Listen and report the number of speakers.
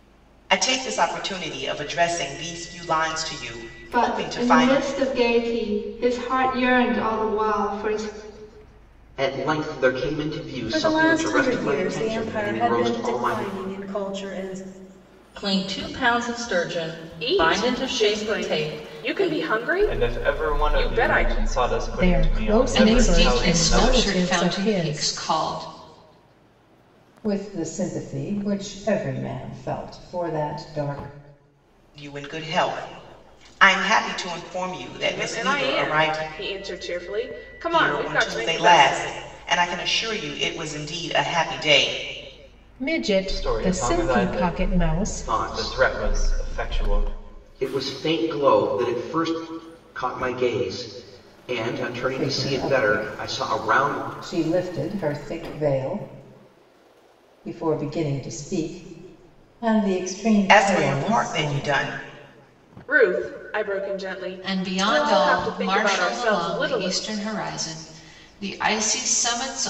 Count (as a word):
ten